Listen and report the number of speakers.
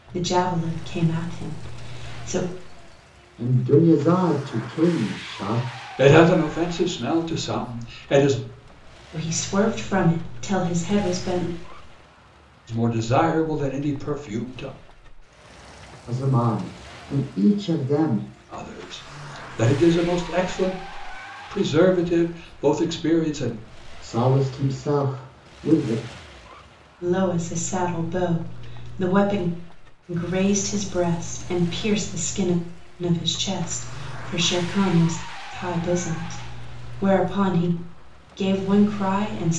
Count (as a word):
three